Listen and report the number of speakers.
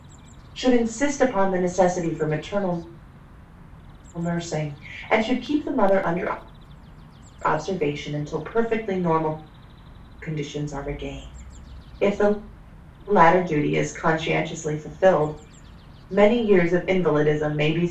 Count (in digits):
1